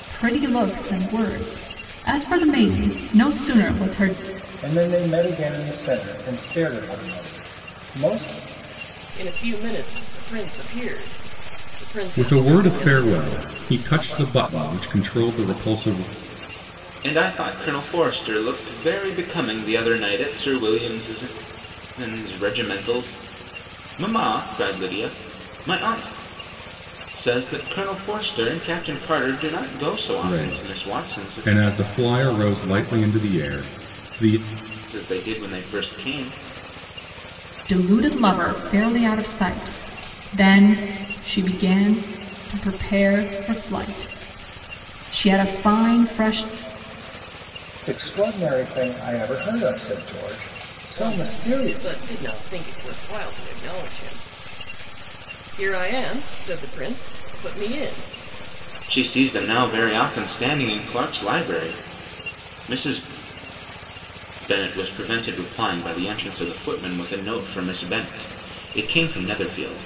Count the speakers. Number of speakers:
5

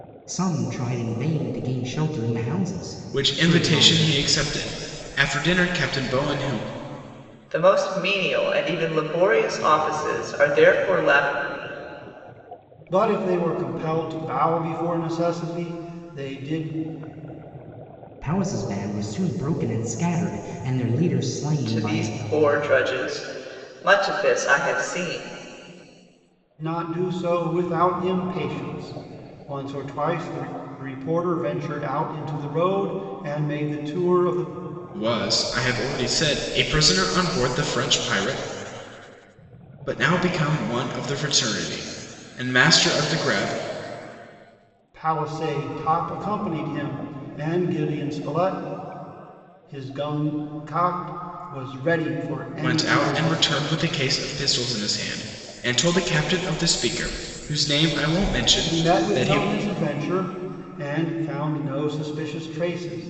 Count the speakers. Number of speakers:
4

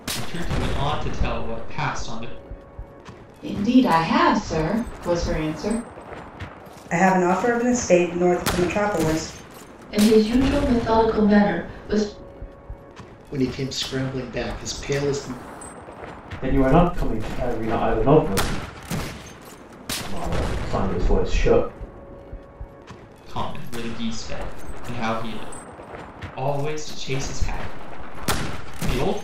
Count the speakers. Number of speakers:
6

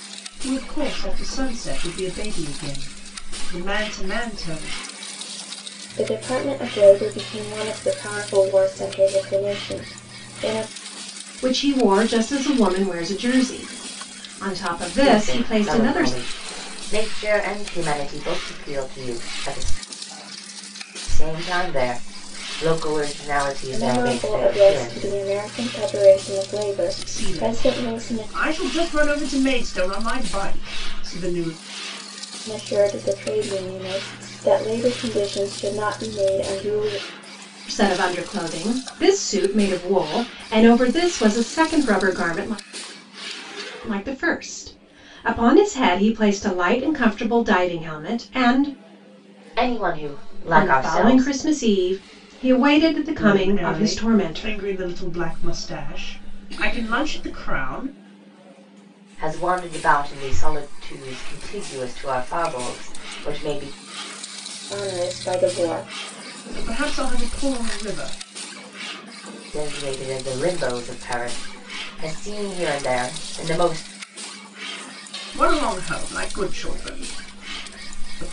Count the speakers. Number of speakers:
4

